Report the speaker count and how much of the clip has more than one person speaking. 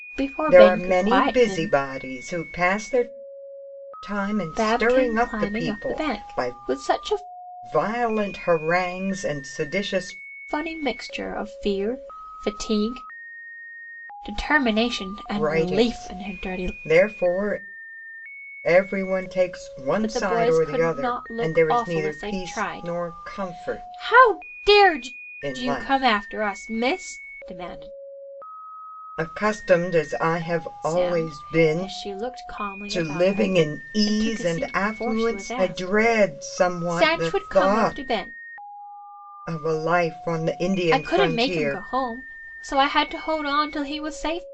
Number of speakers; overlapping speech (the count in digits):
2, about 34%